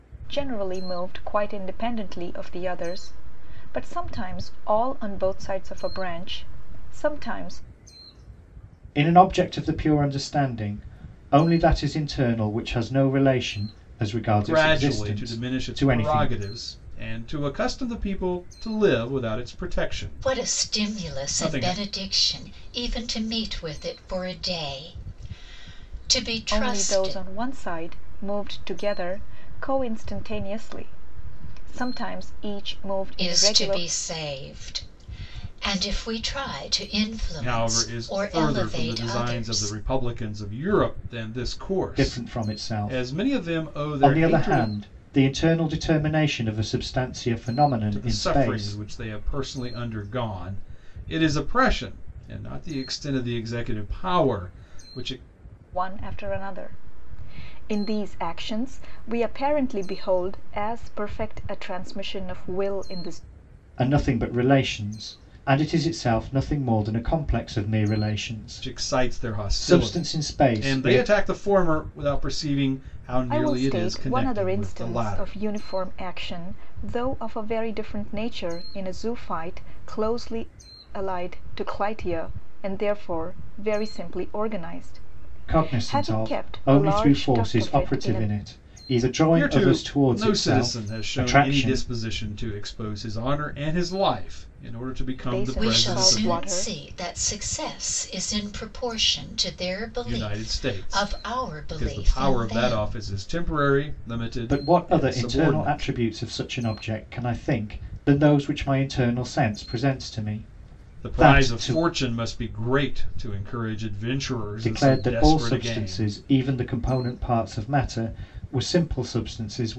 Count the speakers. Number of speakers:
4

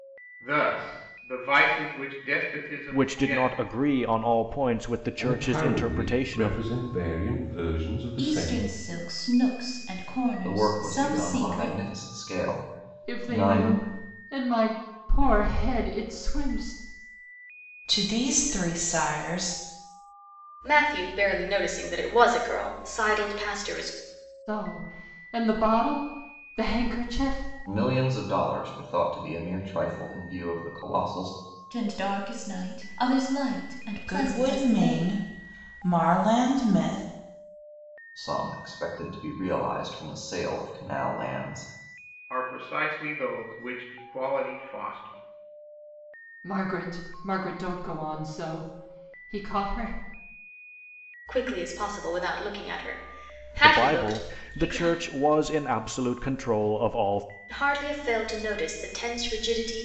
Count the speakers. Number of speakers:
8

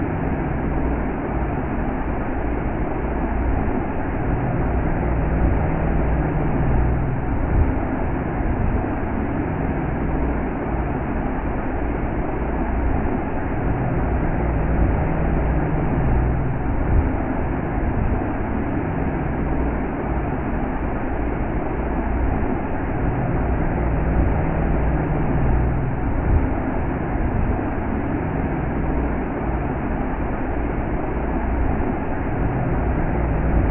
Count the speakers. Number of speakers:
0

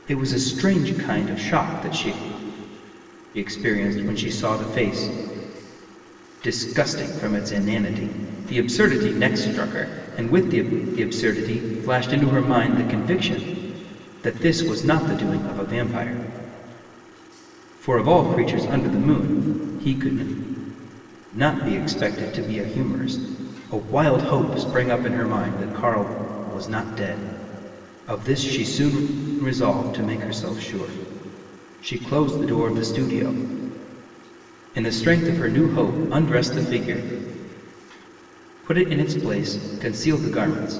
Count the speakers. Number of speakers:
1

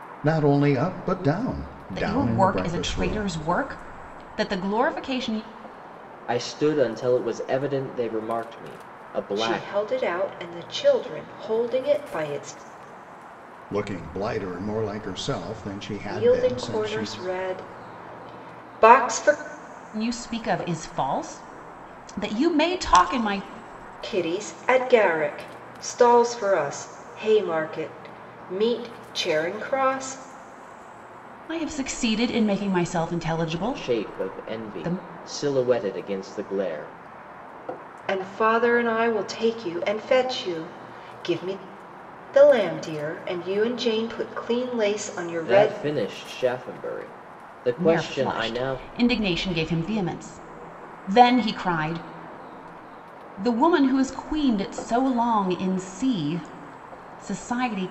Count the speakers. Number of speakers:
4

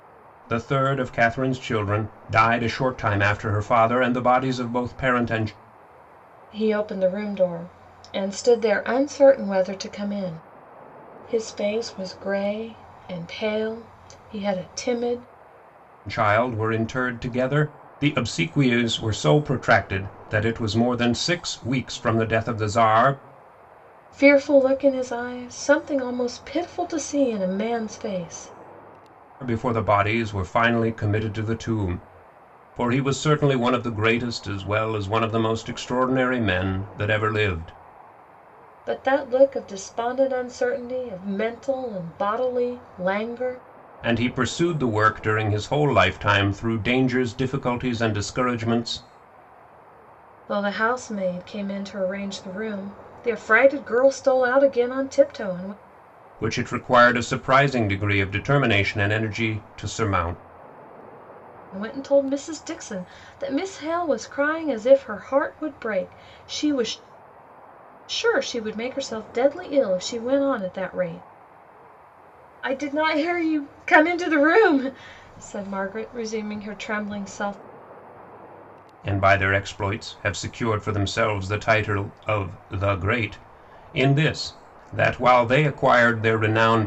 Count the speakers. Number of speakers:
2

